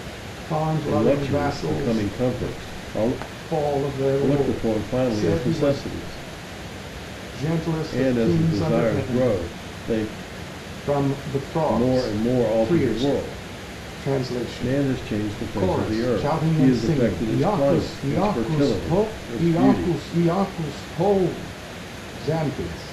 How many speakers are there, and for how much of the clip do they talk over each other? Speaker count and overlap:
2, about 49%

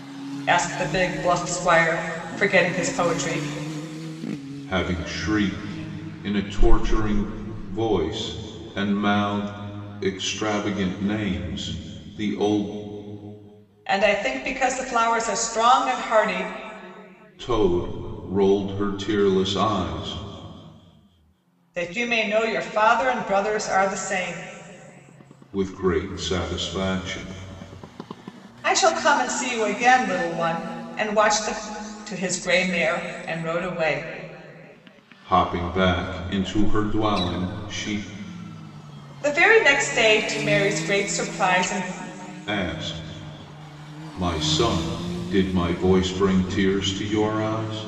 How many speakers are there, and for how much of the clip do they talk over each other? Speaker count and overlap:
2, no overlap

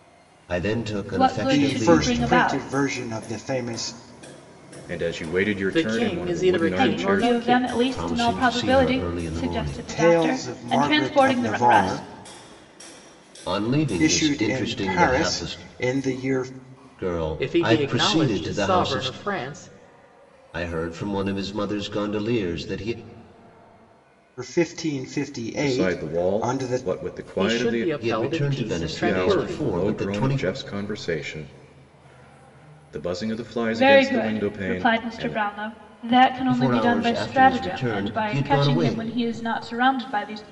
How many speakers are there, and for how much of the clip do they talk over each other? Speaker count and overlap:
5, about 48%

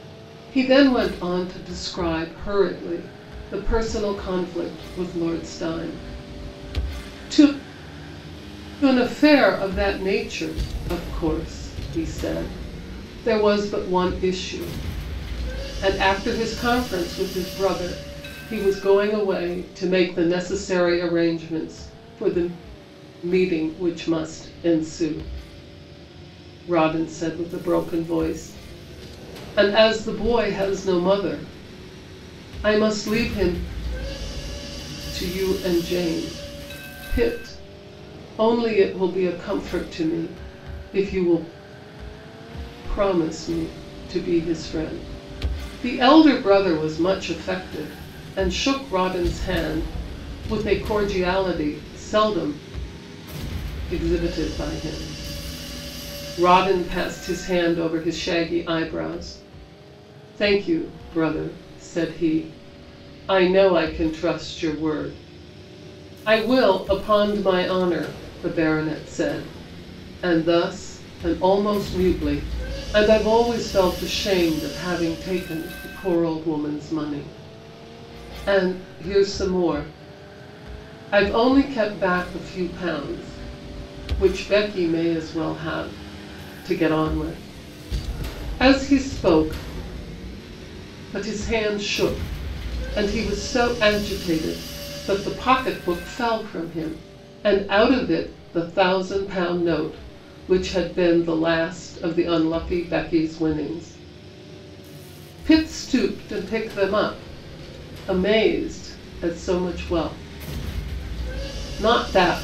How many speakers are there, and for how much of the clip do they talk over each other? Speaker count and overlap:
1, no overlap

